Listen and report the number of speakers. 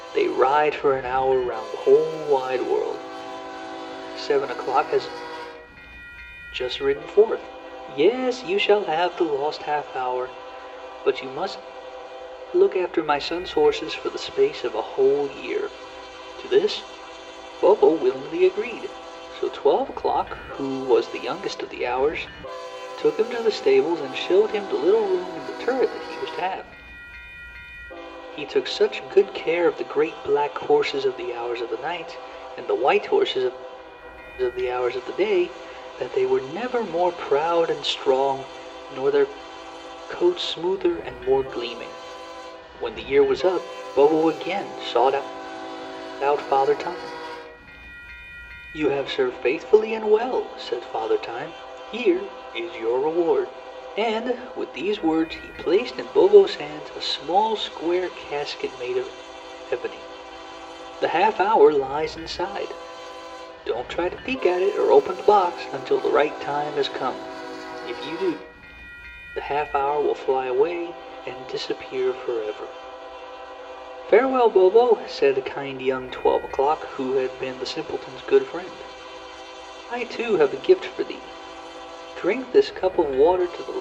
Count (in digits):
1